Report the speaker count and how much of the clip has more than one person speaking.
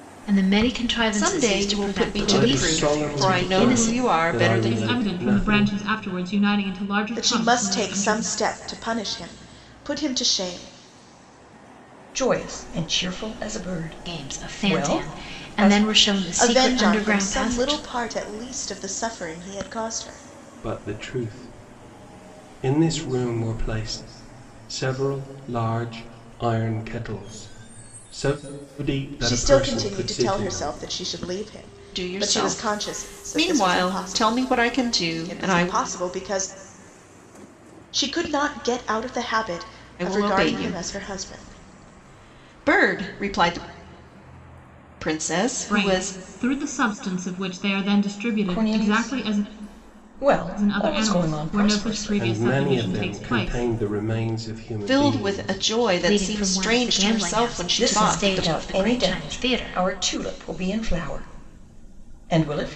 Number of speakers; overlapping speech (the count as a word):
six, about 41%